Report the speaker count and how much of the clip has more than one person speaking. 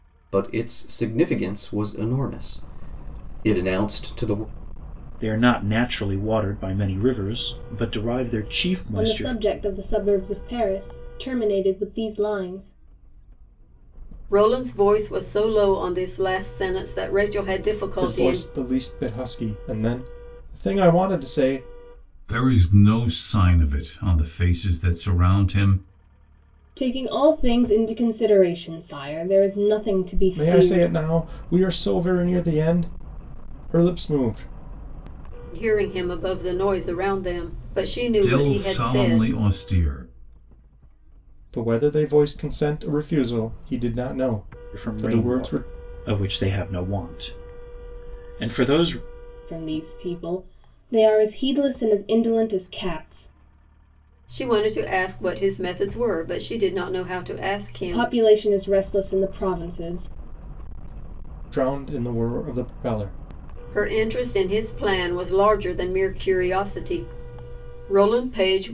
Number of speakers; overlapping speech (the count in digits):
6, about 6%